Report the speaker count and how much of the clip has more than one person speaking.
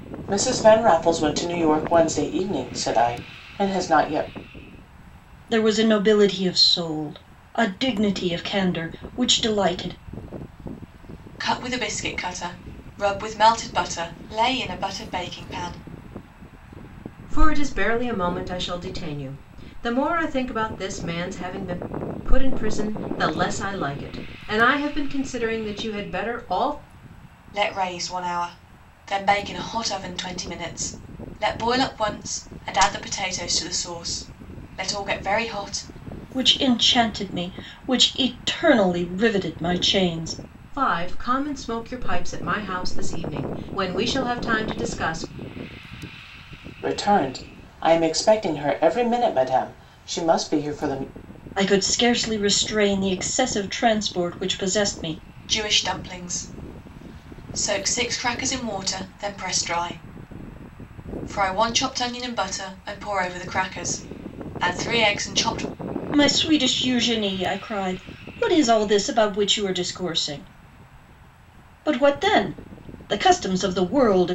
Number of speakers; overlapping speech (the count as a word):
four, no overlap